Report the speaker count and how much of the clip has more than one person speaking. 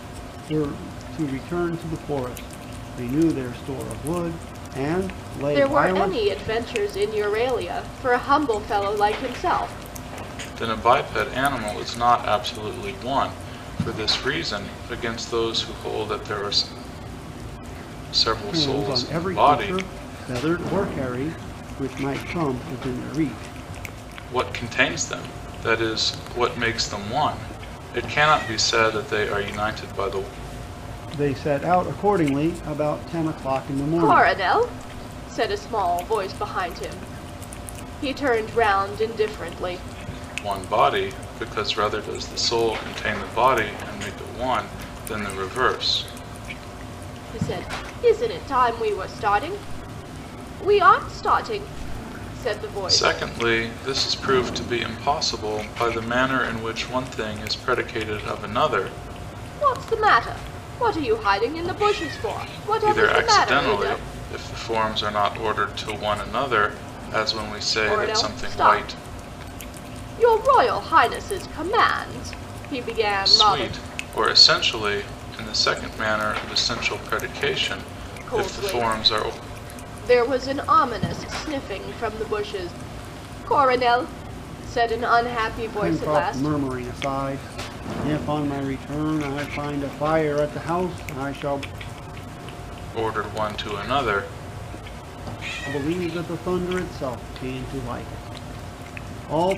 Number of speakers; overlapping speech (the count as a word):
three, about 8%